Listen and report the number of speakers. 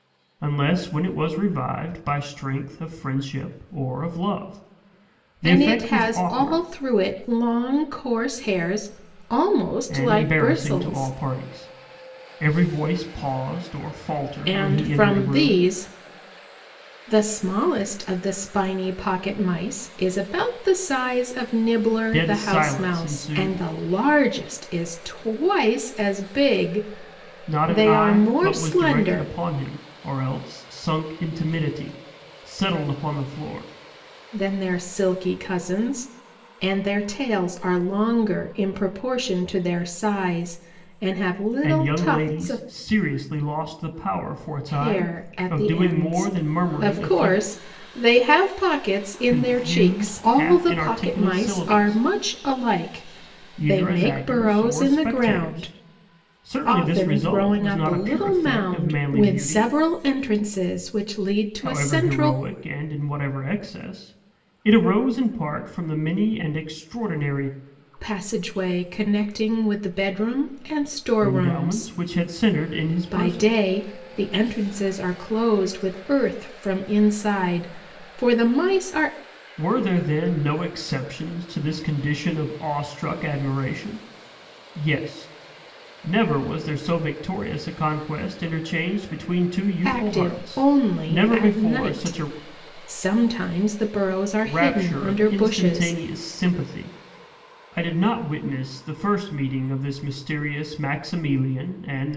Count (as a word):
two